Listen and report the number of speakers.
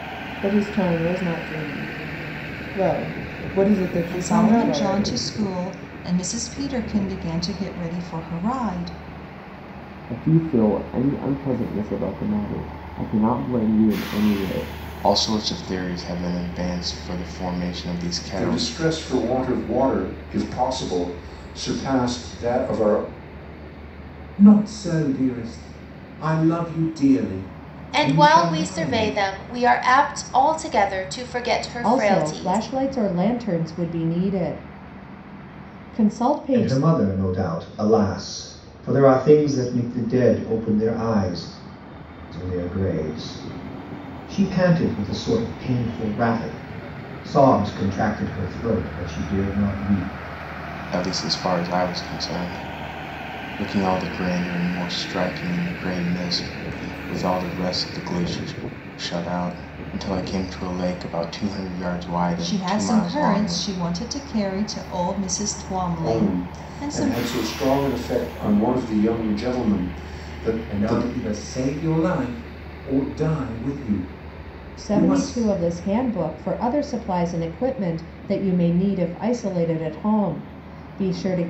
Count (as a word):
nine